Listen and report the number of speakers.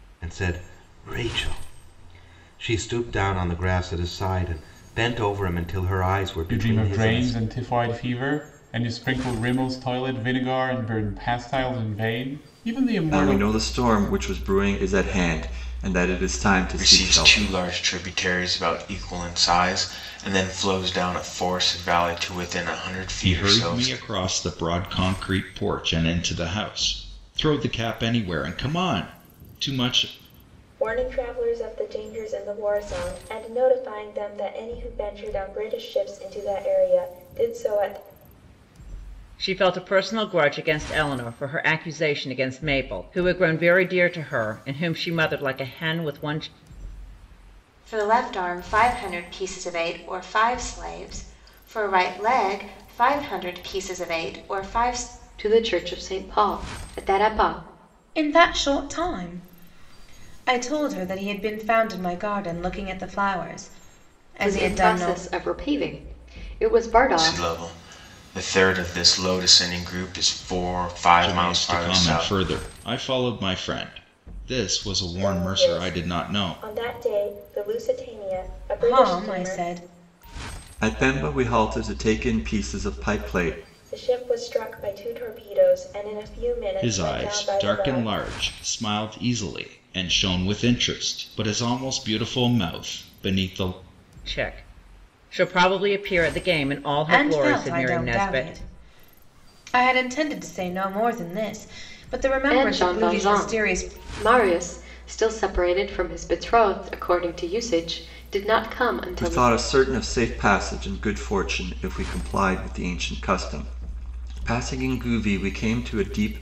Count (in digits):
10